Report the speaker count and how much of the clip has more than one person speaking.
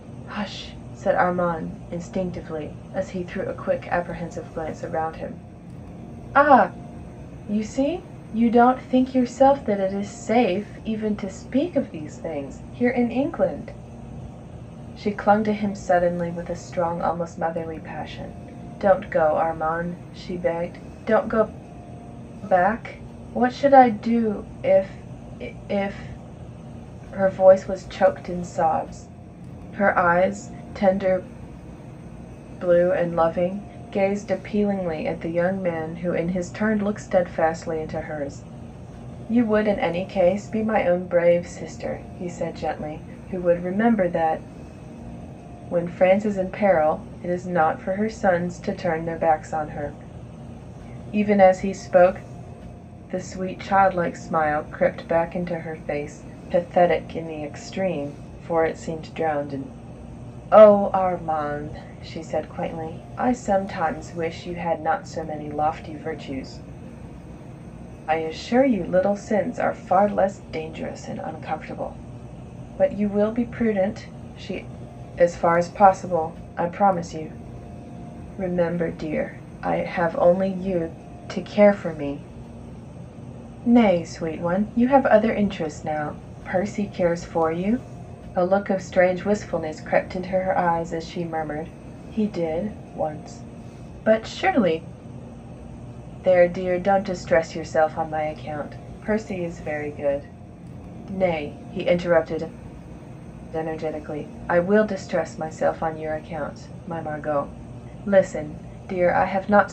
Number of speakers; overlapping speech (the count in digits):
1, no overlap